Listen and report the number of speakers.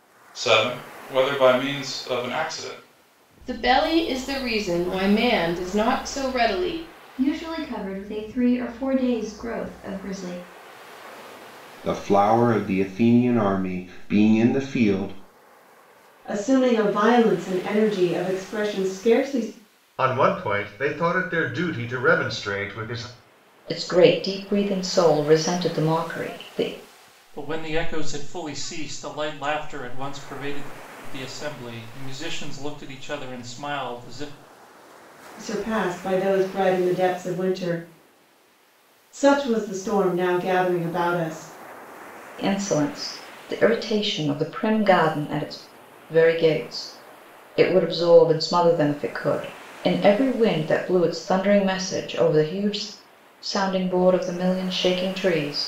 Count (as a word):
eight